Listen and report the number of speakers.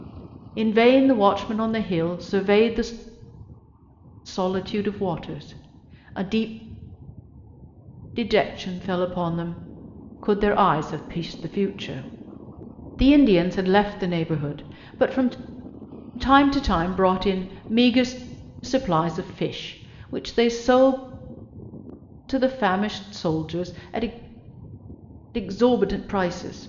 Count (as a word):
one